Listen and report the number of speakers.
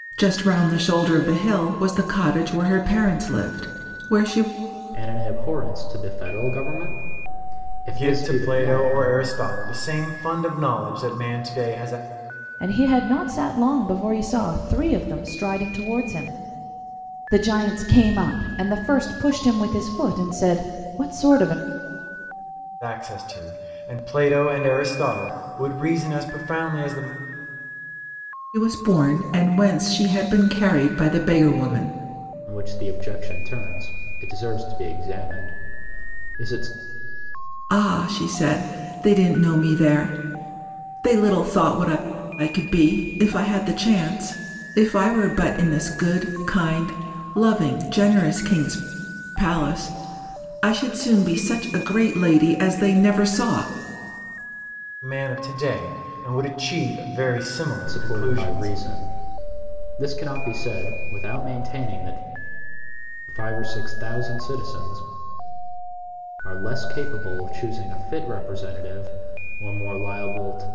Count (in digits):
4